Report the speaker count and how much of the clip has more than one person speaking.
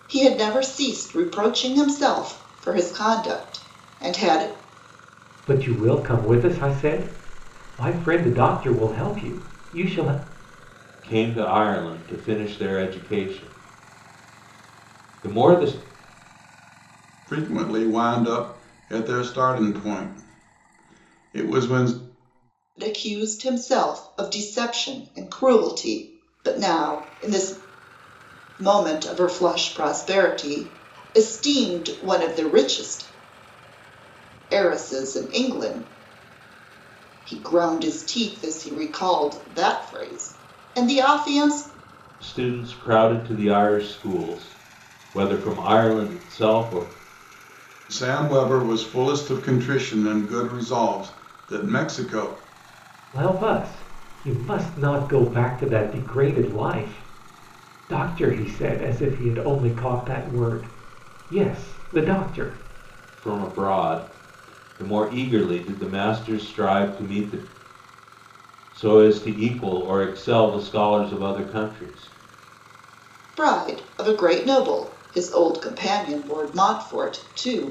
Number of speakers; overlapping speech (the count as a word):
four, no overlap